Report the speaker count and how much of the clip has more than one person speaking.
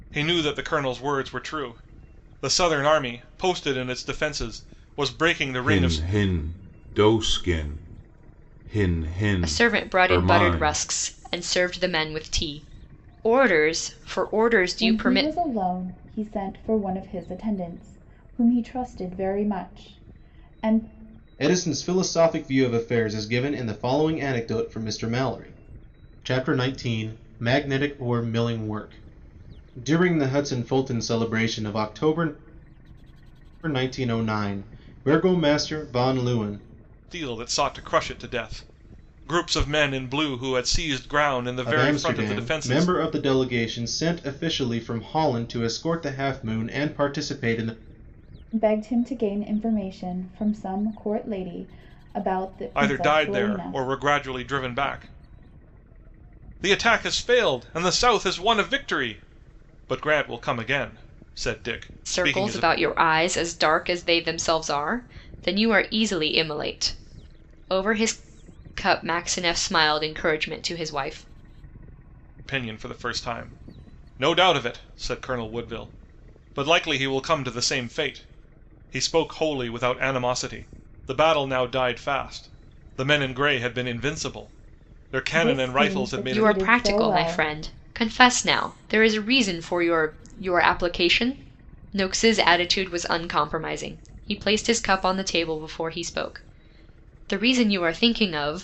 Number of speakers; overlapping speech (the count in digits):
5, about 8%